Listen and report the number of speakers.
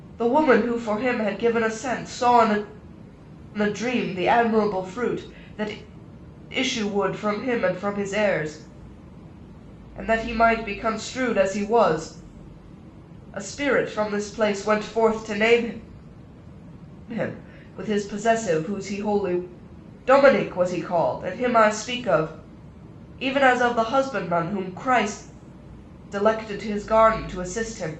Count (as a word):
one